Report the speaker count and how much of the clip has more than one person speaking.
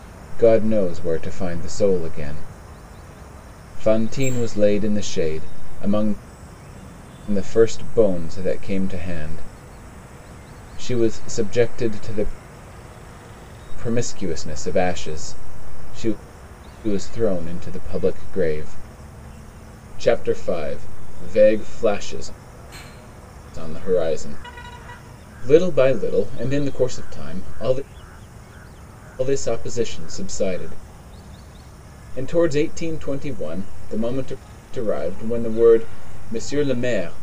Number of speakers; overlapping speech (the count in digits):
1, no overlap